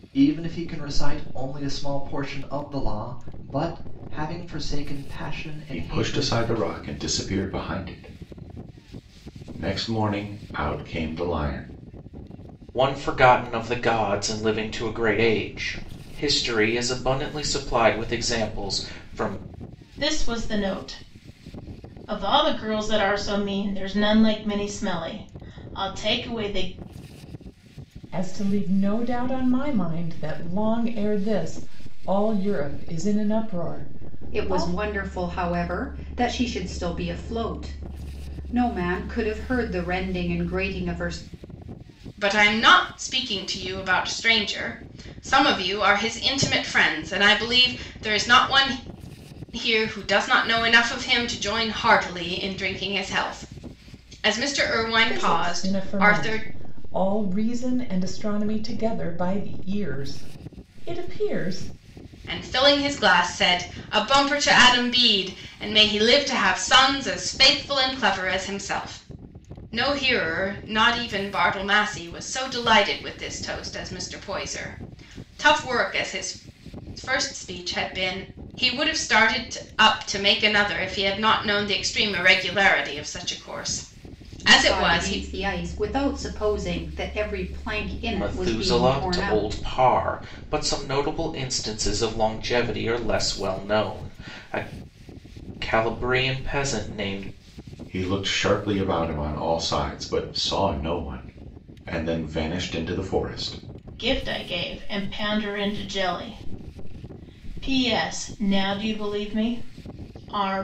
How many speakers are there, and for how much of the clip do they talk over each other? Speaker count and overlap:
7, about 5%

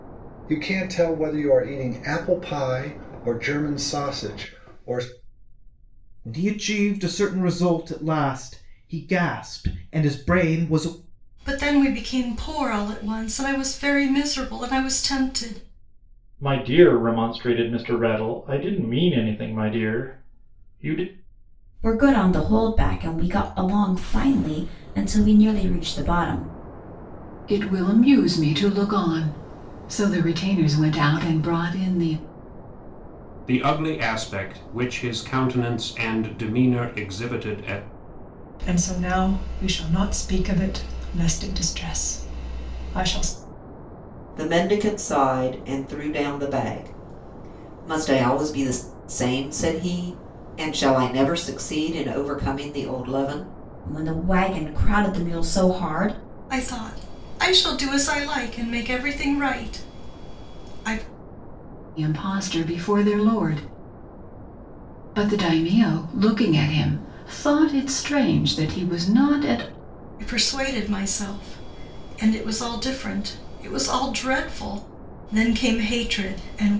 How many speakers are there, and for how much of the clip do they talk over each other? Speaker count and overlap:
9, no overlap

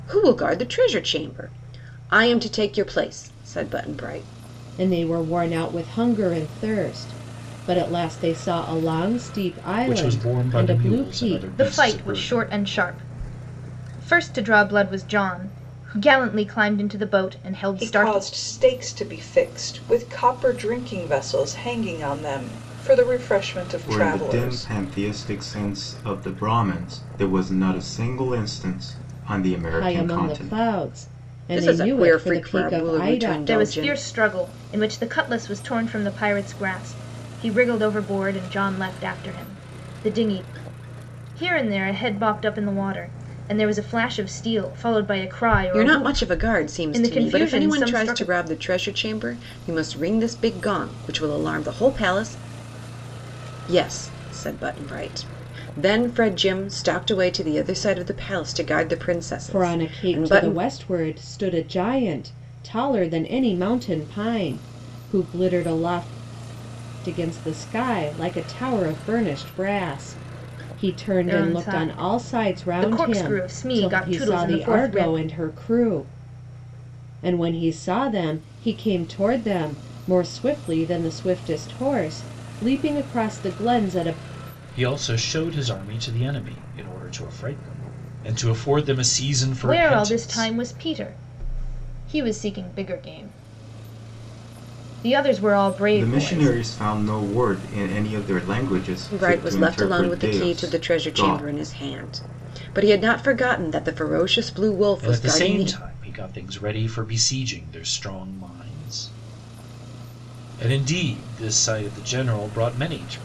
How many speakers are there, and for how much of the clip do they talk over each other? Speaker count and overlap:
6, about 18%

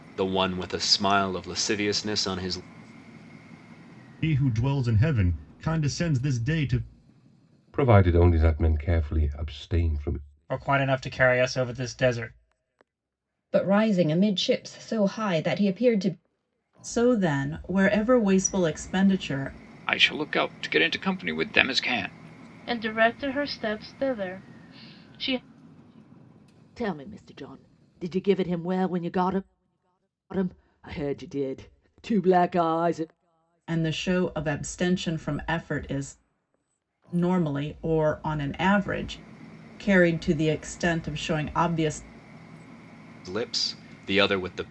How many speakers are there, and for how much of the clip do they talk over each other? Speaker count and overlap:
9, no overlap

